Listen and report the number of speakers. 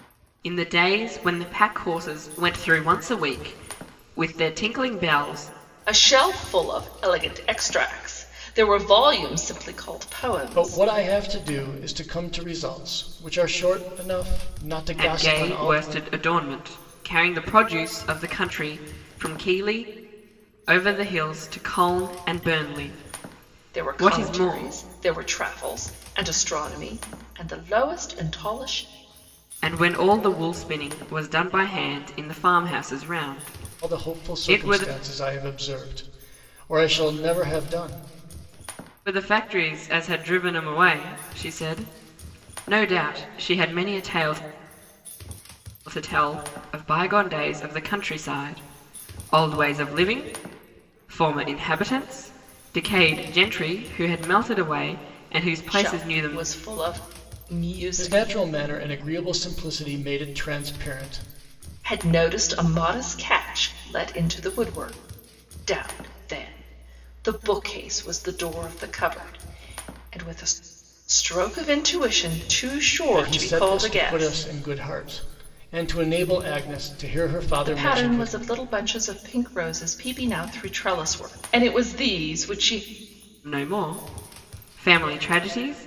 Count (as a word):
three